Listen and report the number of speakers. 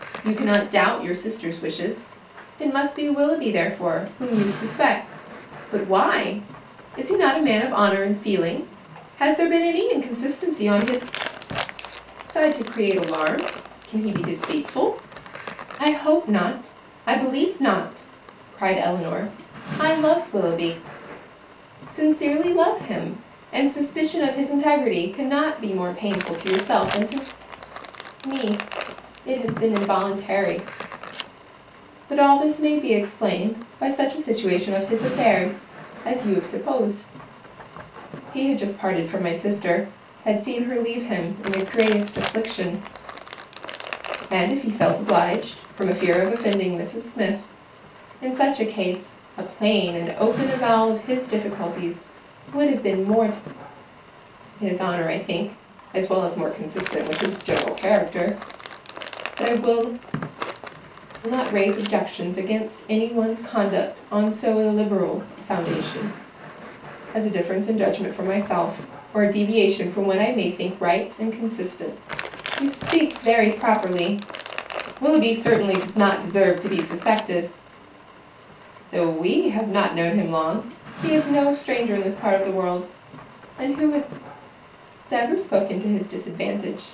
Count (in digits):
1